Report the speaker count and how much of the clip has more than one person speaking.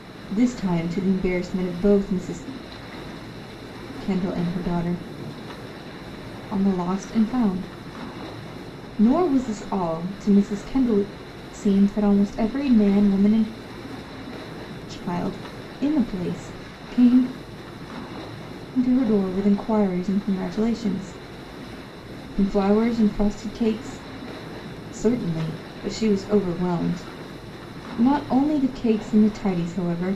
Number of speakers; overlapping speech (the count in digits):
1, no overlap